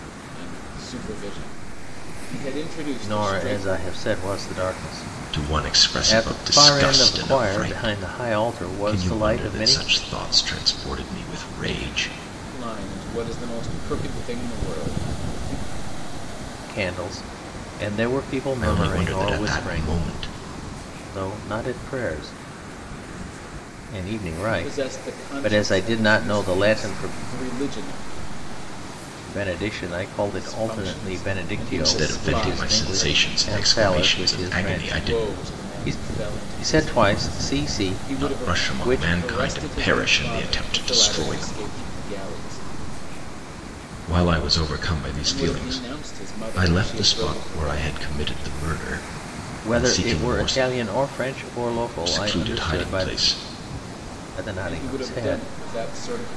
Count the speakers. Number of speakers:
three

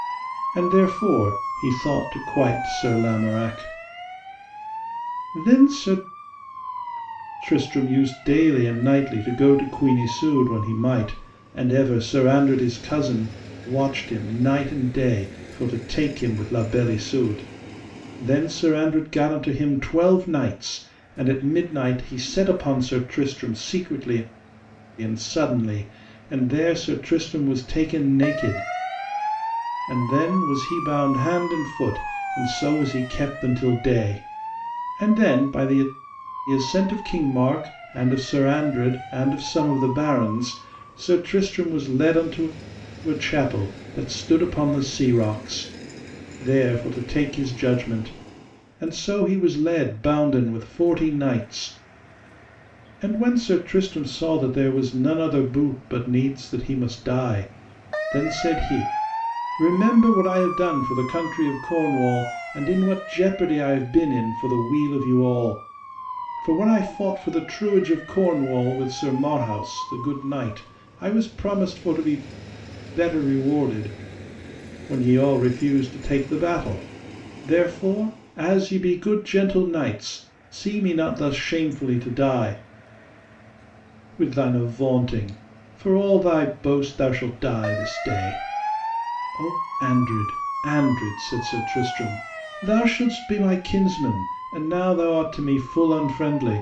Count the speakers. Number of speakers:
one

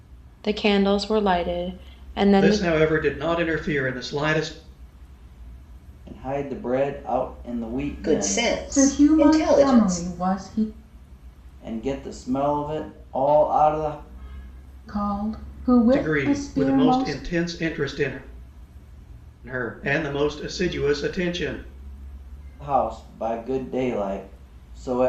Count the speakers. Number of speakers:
five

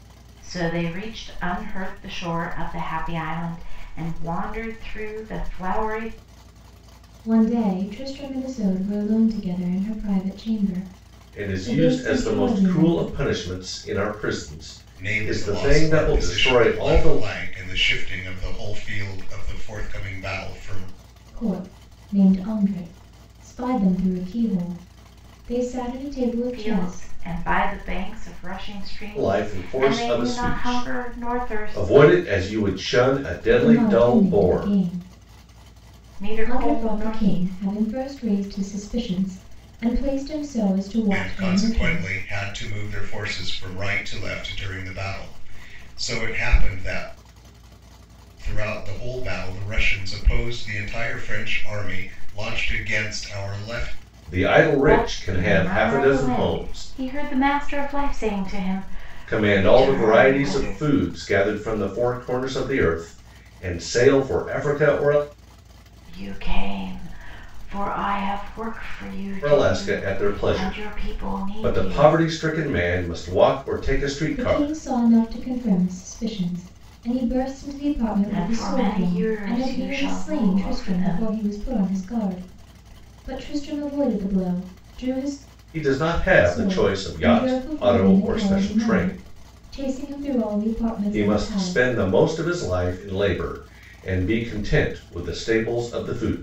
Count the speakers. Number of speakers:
four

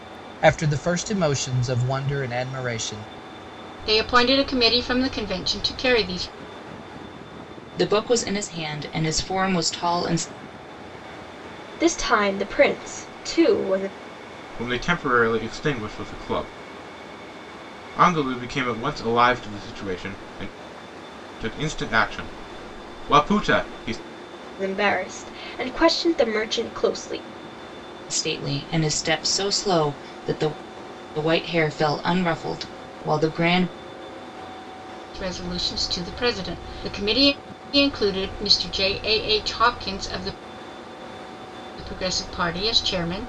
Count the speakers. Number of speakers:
five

